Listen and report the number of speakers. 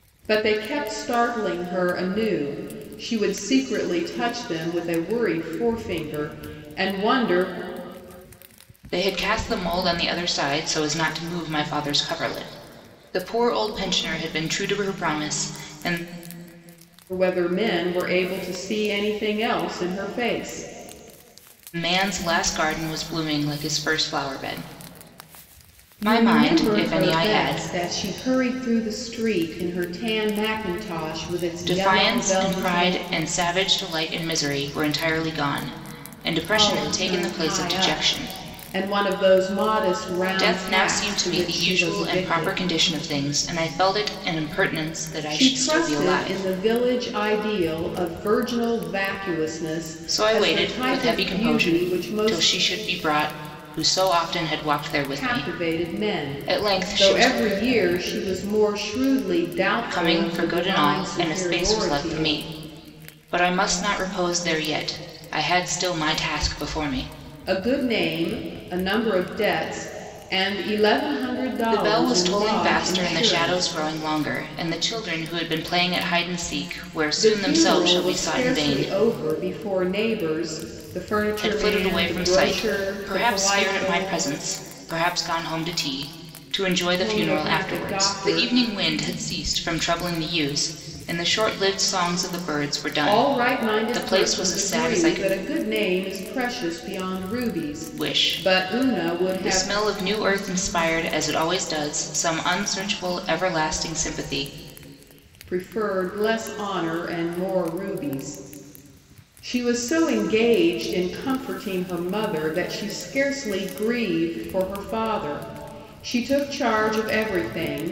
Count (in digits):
2